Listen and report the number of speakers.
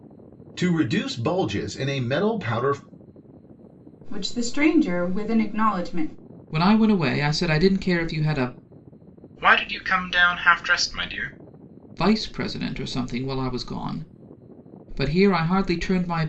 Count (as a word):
four